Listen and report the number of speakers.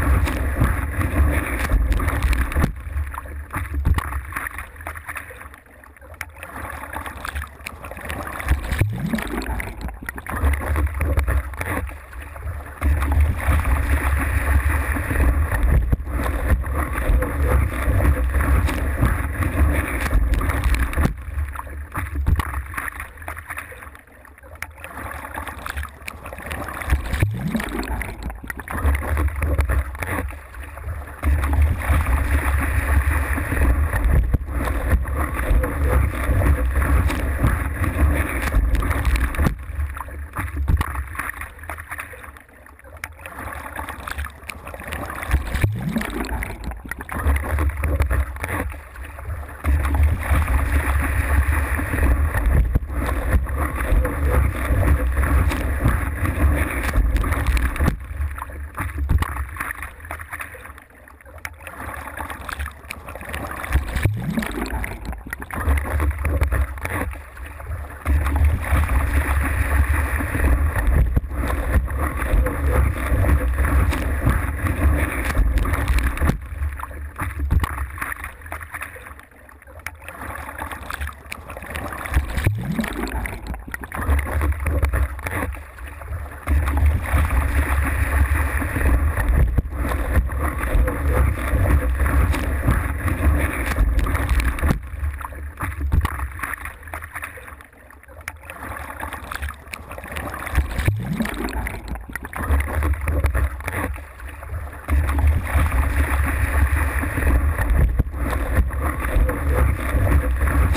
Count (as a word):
zero